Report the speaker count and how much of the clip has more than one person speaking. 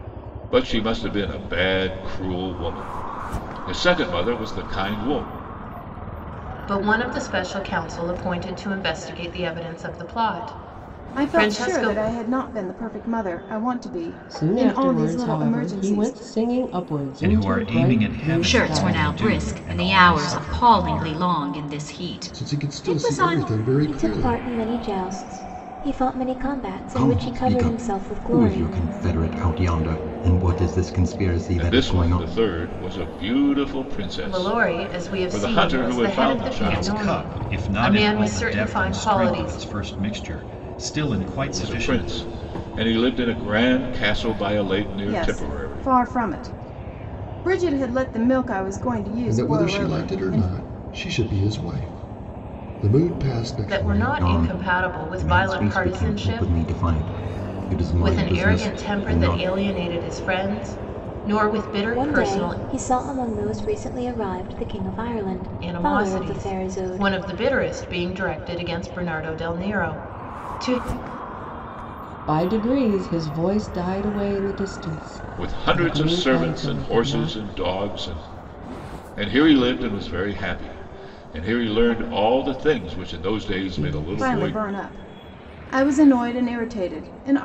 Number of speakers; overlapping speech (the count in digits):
9, about 34%